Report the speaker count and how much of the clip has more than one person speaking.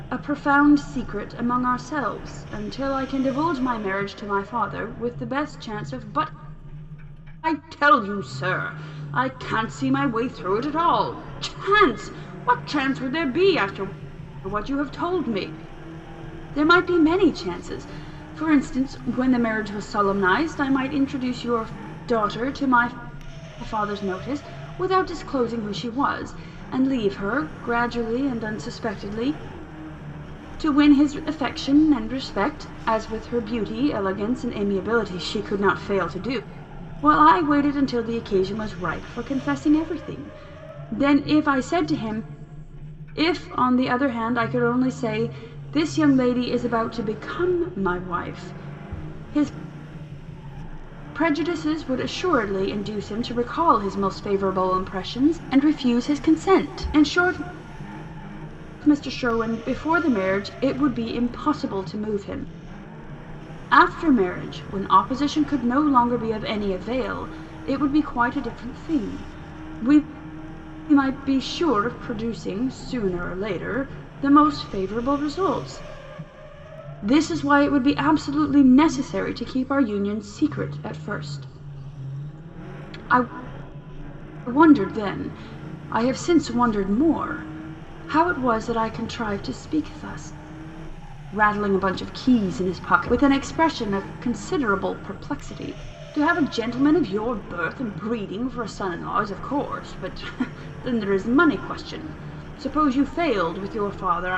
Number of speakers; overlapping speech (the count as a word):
one, no overlap